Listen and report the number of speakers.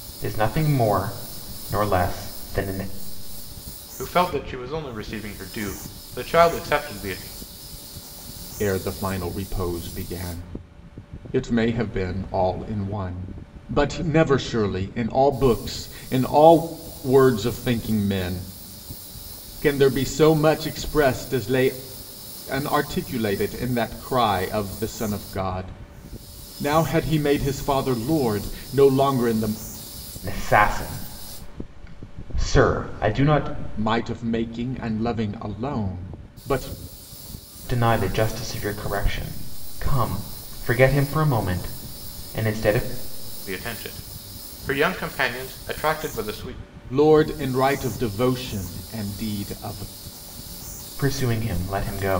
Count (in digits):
3